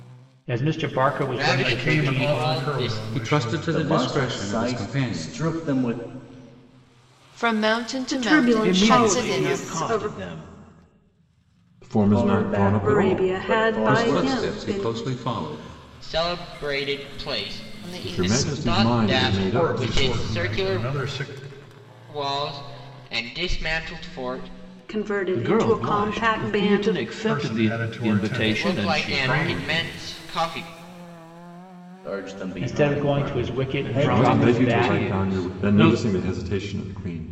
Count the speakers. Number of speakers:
9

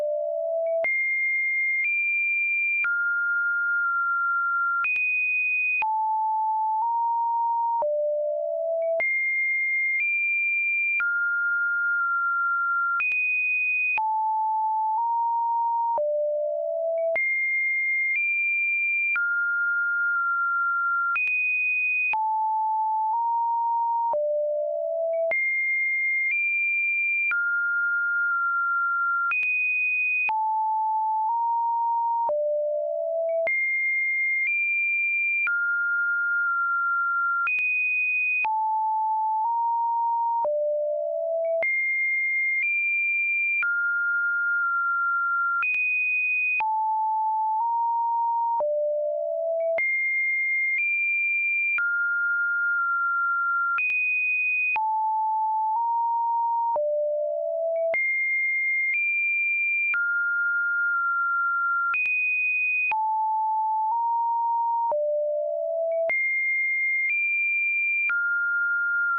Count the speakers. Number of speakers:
0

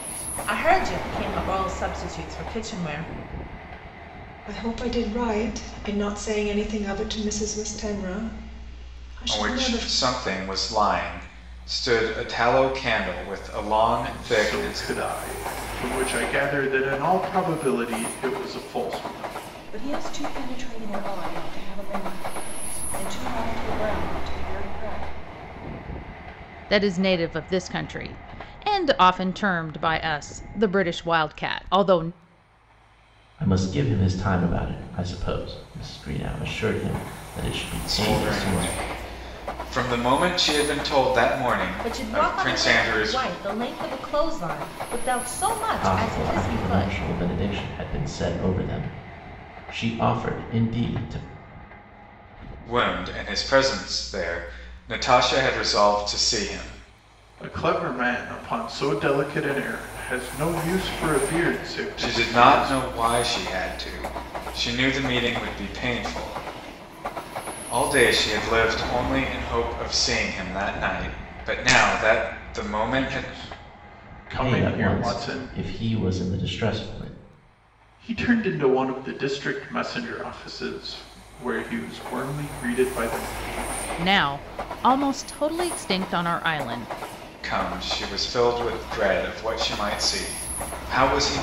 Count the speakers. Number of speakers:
7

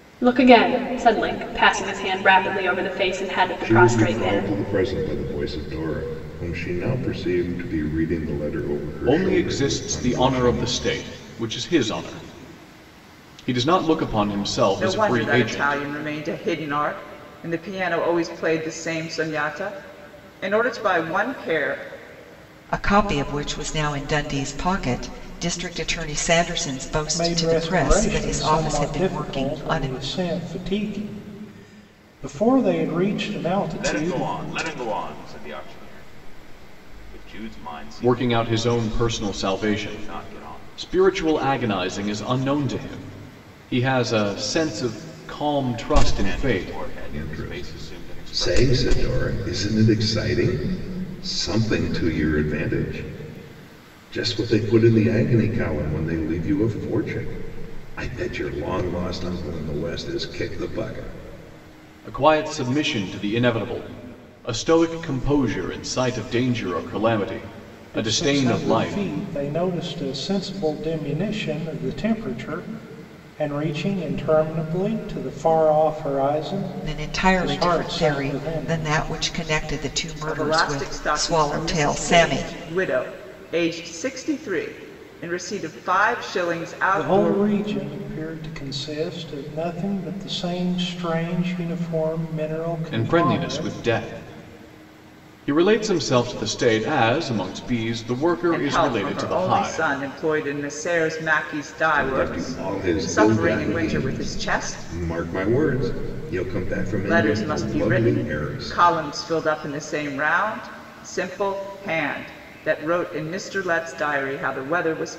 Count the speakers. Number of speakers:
7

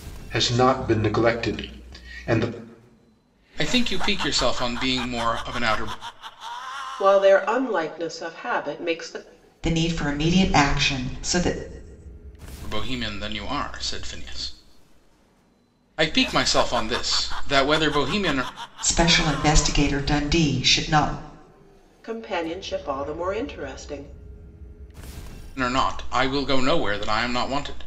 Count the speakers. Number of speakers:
4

